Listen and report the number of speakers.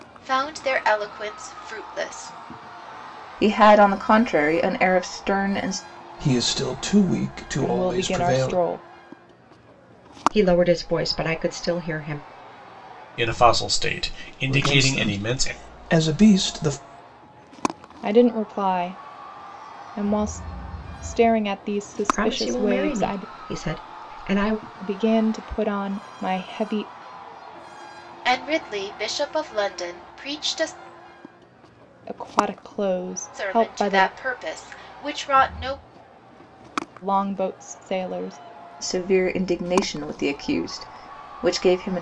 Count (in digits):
6